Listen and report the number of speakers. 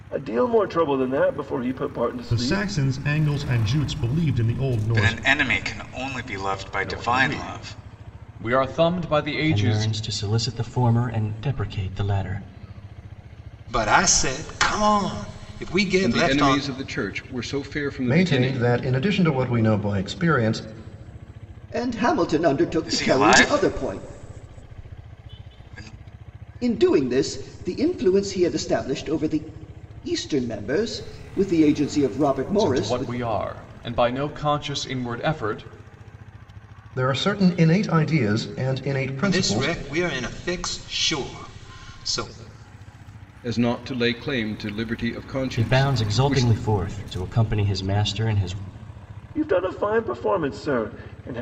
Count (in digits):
9